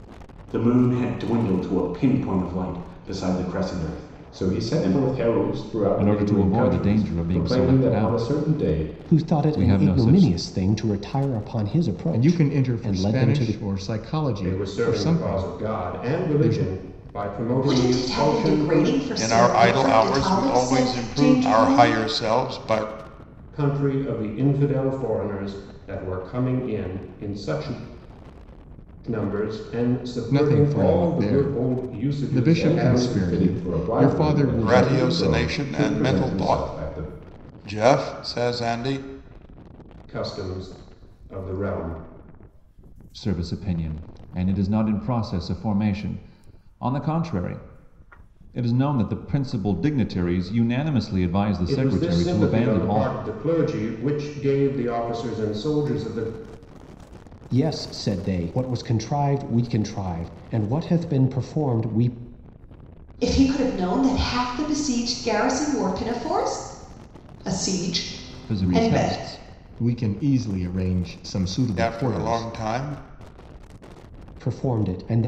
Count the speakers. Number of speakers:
8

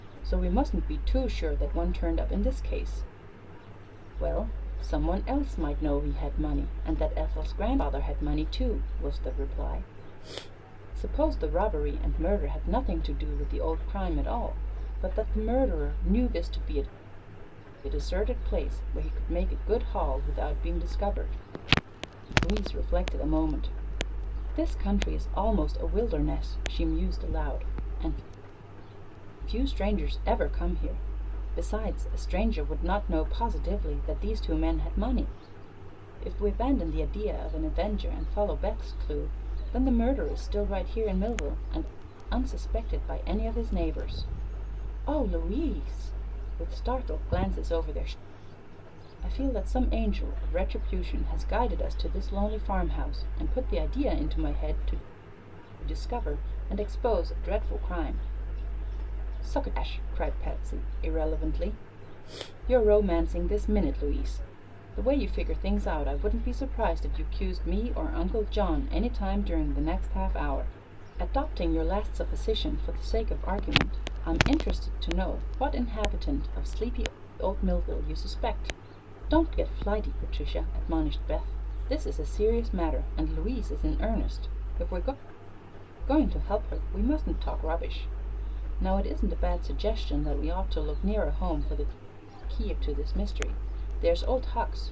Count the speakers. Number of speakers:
1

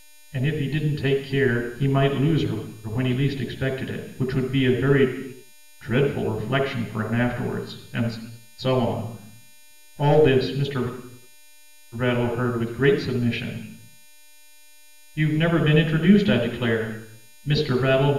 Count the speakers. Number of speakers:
1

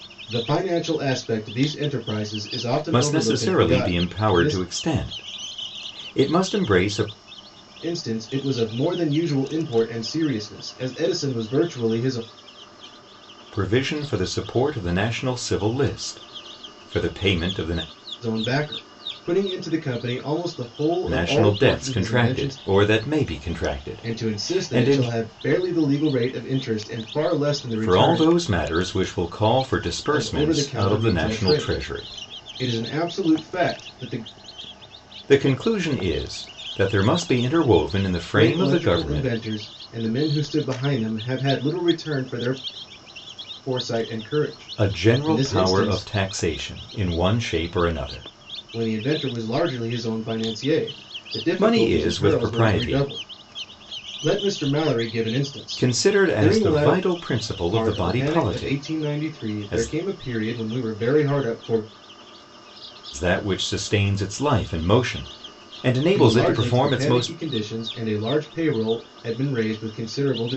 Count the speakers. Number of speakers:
2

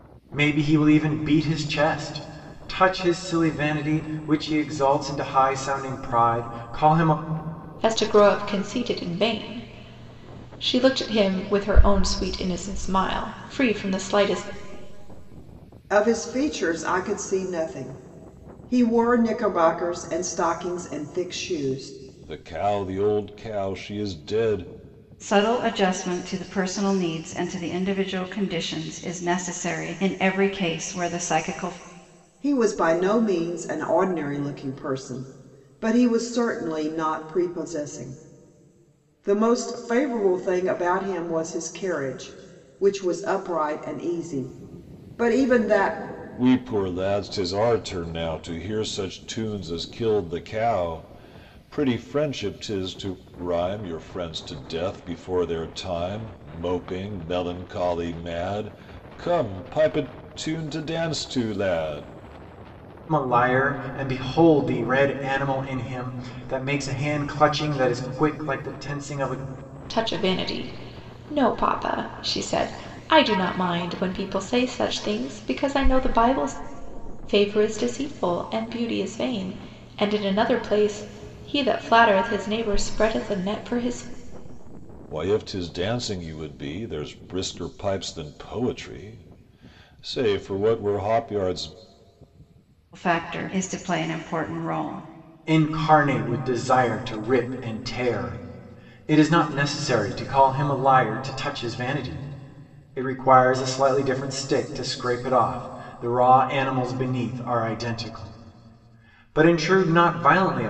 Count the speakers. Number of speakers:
5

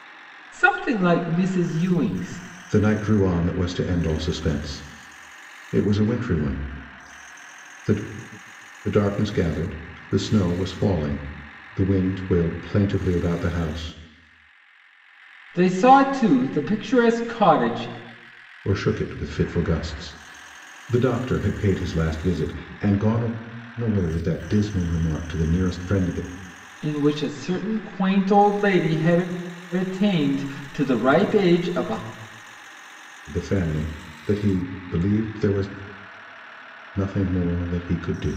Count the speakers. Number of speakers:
2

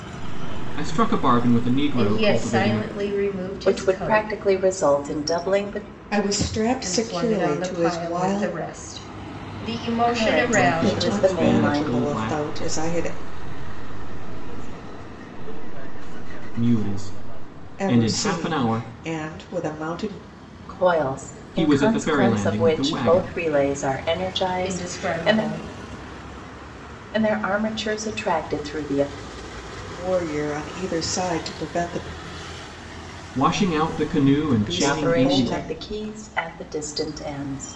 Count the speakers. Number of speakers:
5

